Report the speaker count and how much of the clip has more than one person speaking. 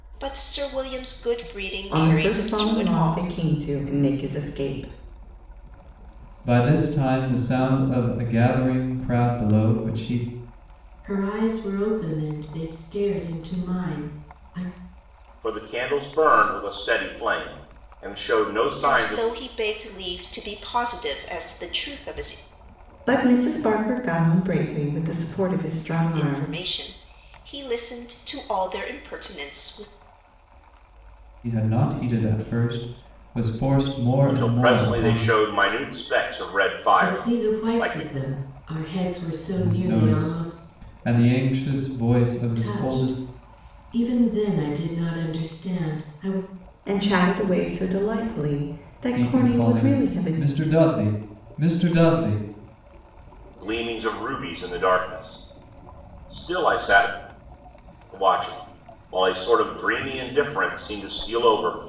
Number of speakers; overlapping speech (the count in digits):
5, about 12%